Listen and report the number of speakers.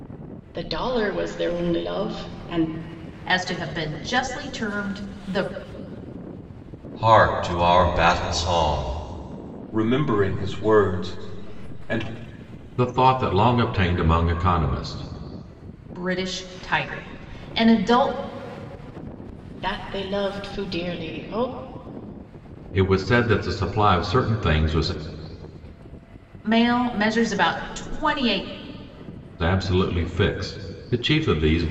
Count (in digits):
5